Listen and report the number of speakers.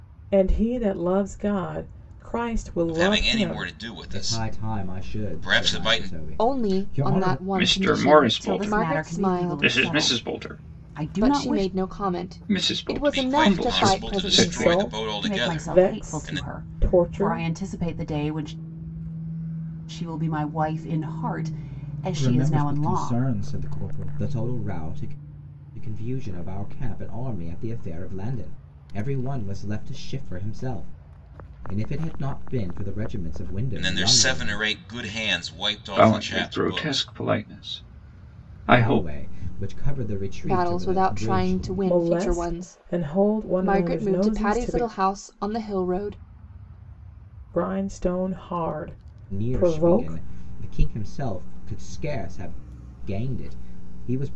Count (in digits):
6